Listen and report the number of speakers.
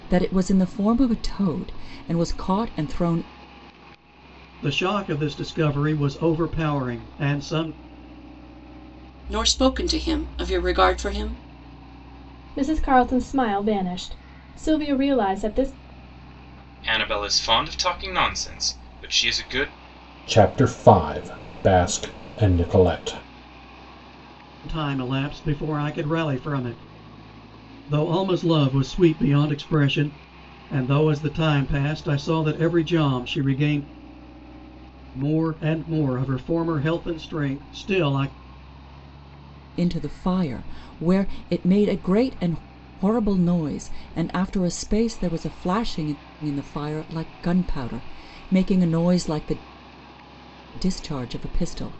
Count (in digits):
6